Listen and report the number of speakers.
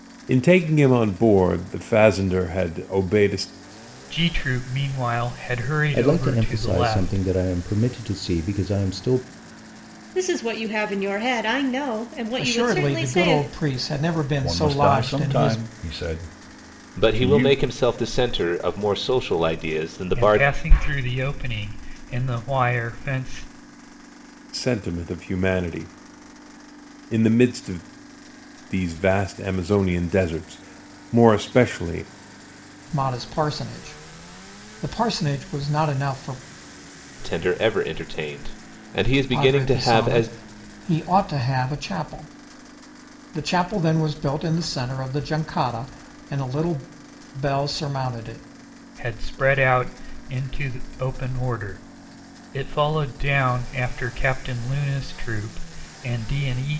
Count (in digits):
7